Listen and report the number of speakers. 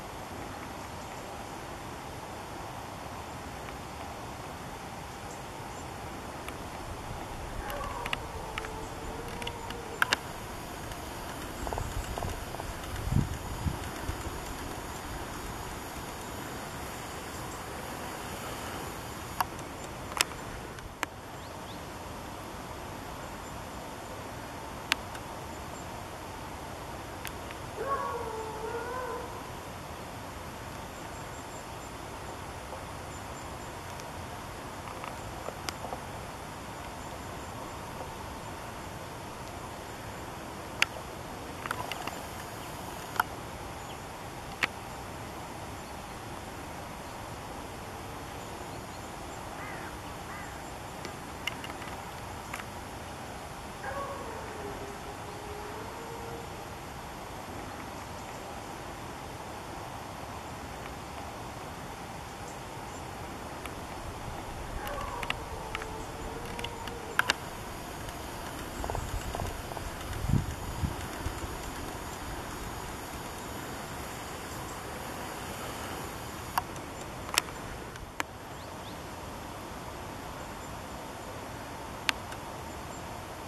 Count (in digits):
0